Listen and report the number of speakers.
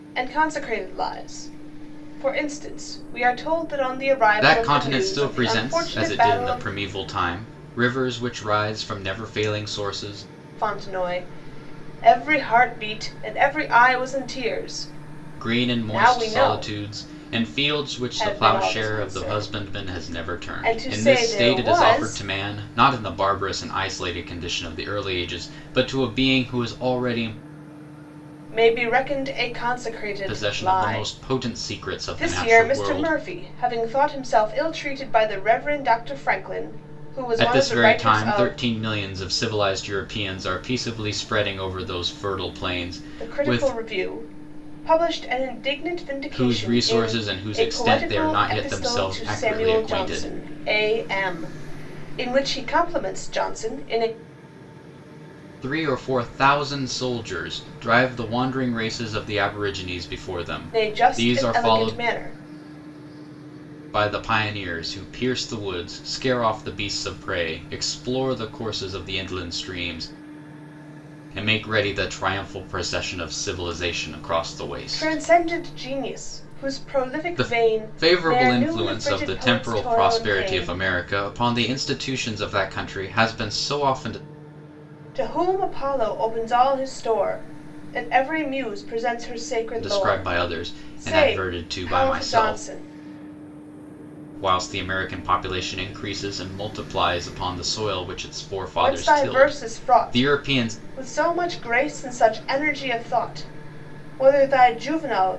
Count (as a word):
two